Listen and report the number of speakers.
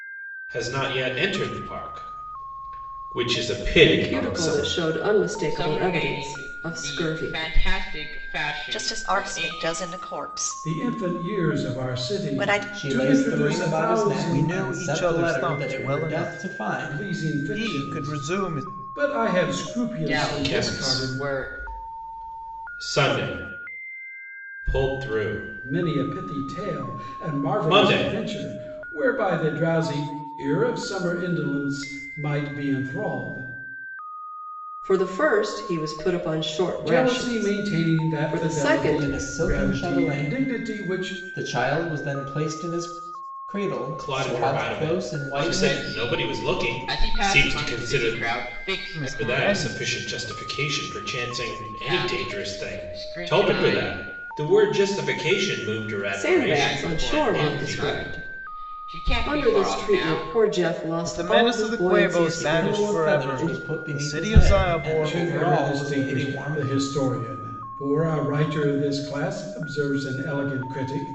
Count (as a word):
seven